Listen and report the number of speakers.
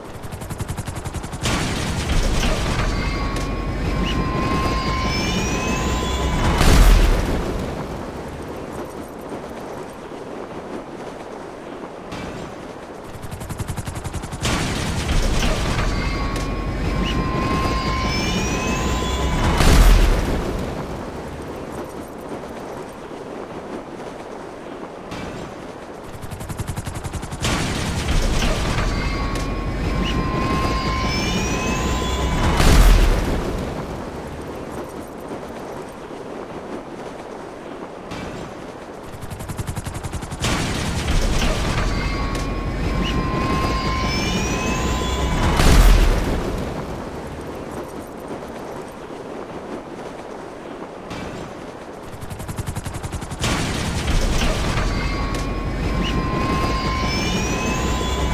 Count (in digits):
0